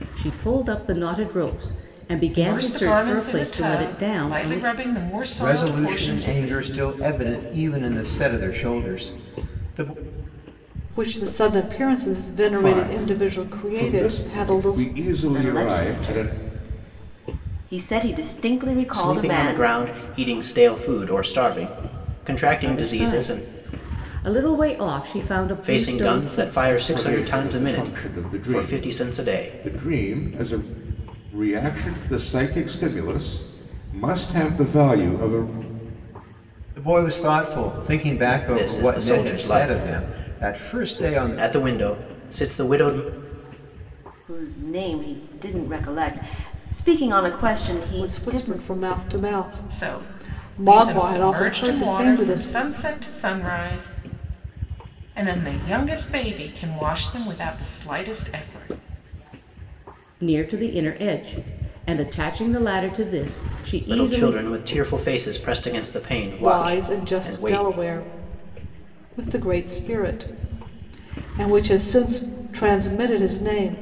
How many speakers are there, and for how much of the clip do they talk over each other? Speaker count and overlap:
7, about 29%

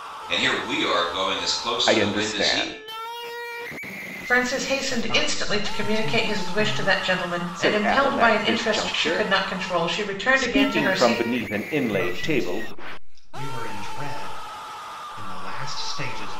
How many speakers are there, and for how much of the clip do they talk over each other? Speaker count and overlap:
4, about 39%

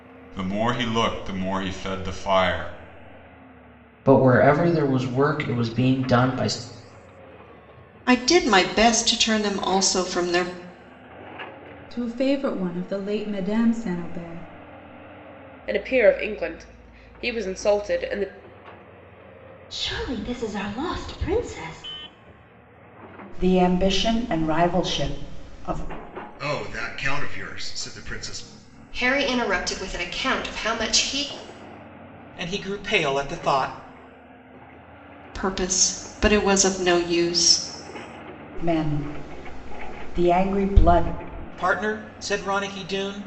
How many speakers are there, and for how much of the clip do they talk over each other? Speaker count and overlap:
10, no overlap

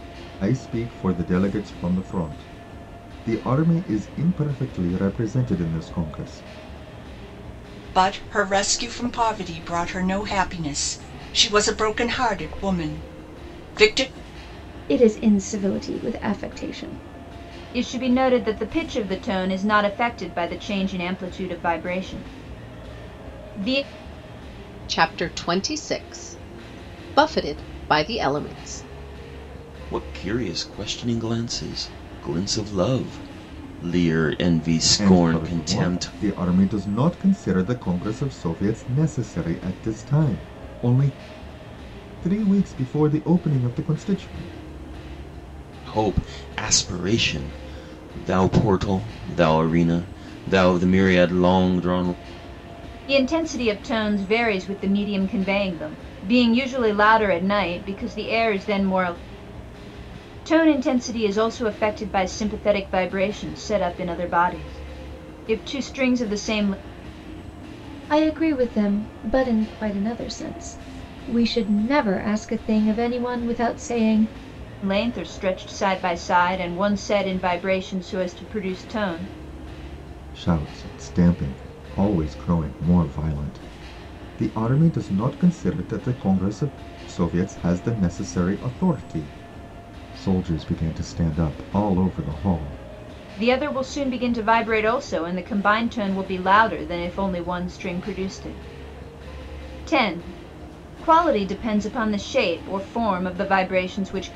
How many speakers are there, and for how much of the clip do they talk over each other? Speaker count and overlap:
6, about 1%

